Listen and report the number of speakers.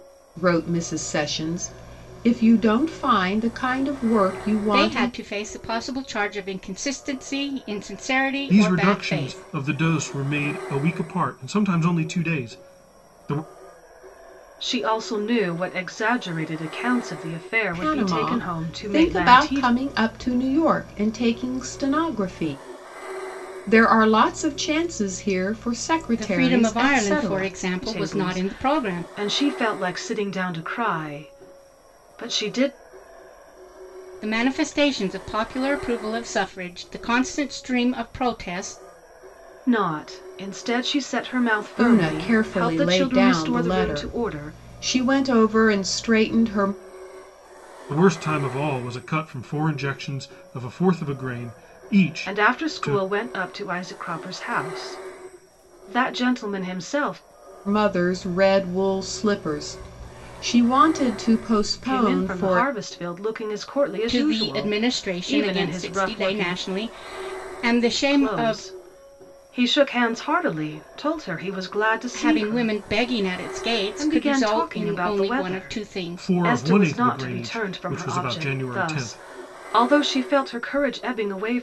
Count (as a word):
four